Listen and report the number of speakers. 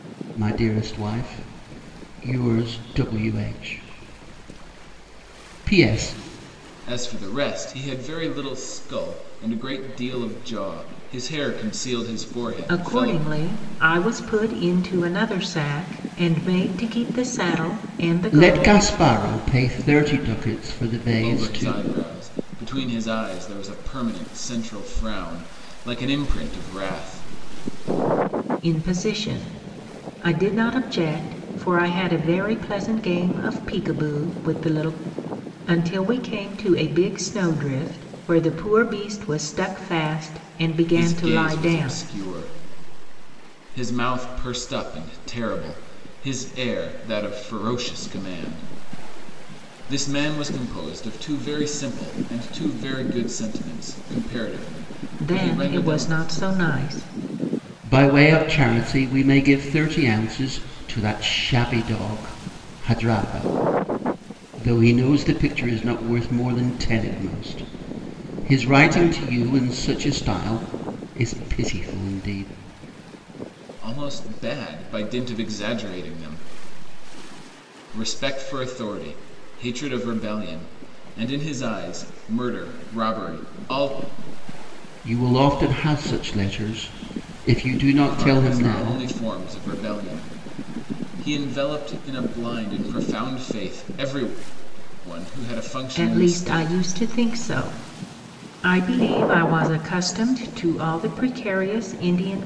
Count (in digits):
3